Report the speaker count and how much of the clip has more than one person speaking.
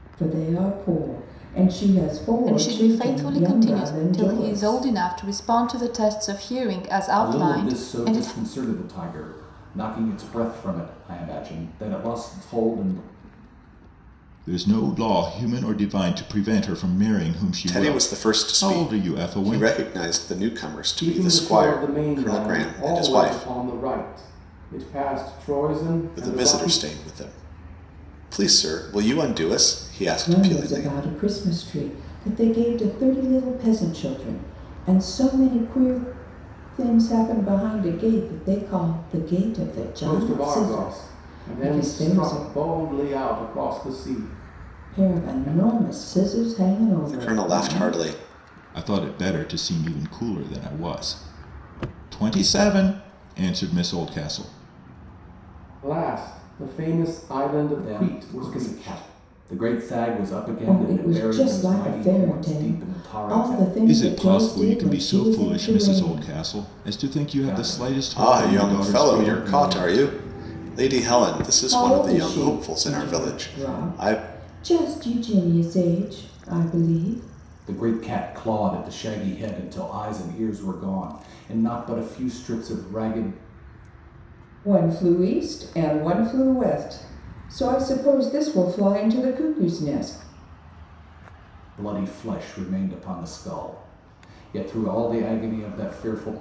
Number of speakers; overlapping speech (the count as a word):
six, about 27%